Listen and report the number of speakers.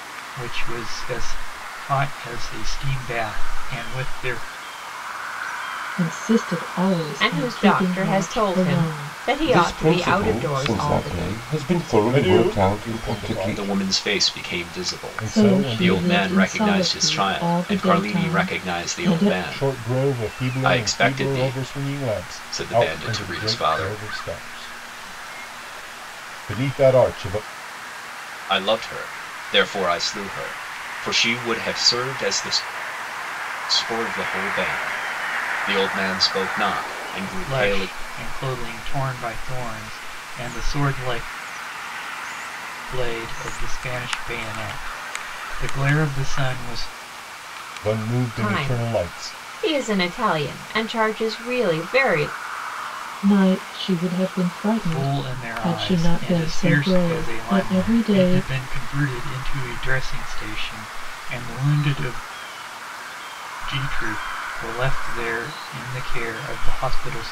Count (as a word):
six